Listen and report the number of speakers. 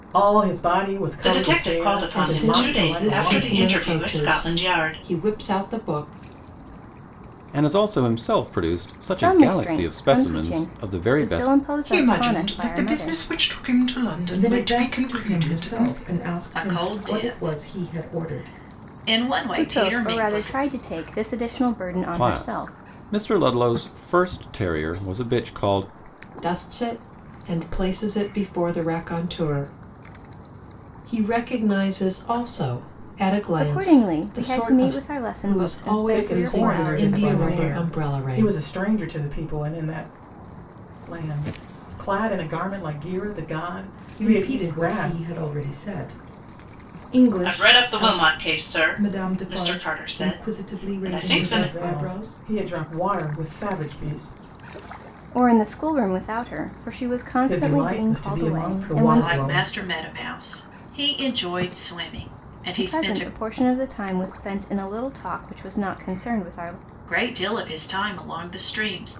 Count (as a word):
eight